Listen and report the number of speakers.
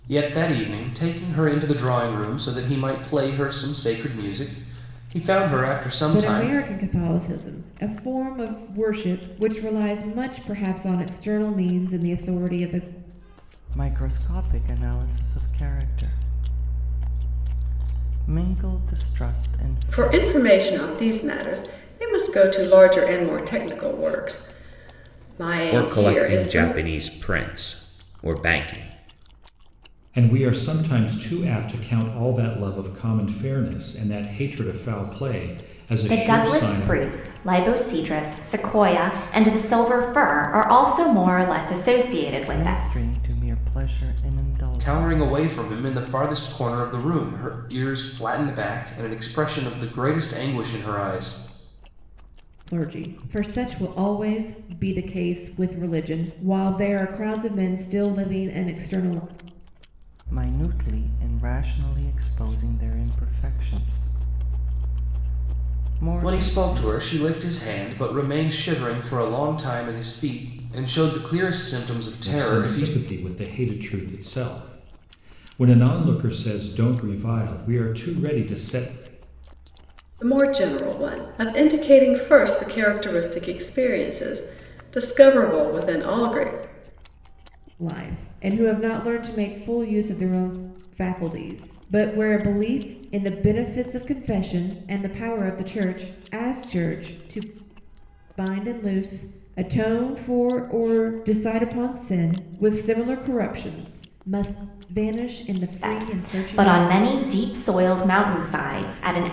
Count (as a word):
seven